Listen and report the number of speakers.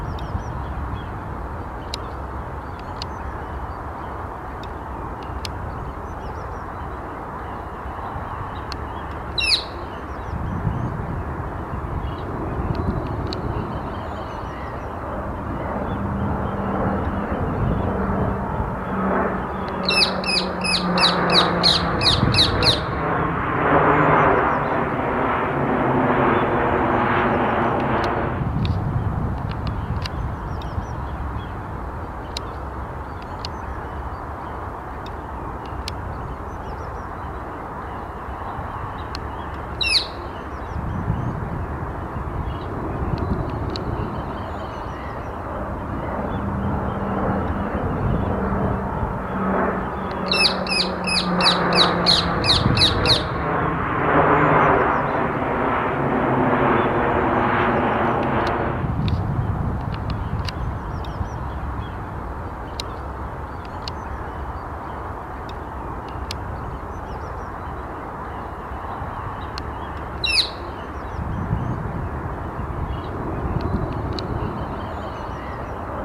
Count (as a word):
zero